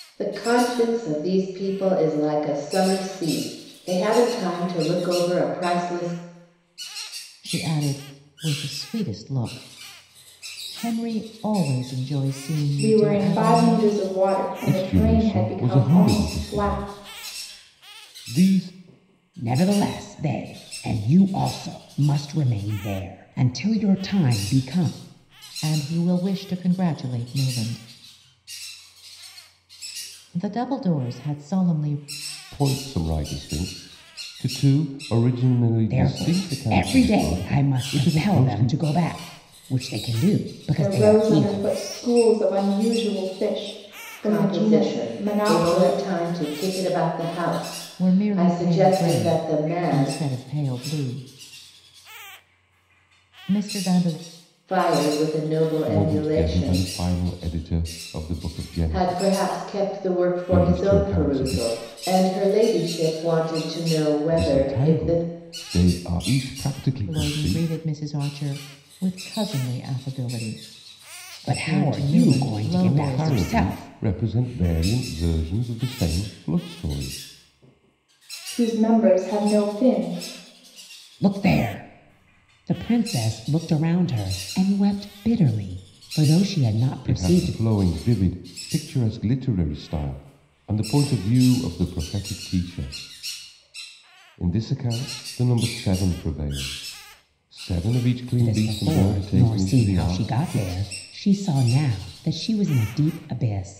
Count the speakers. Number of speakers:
five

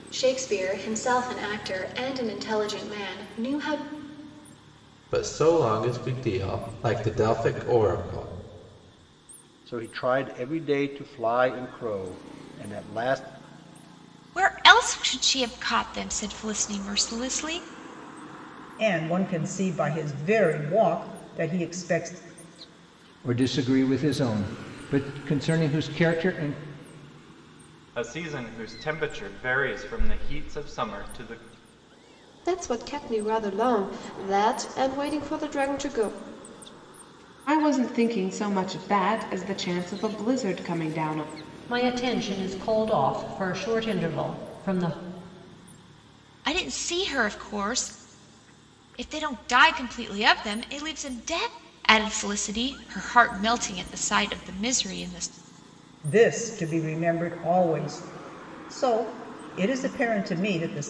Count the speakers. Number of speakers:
ten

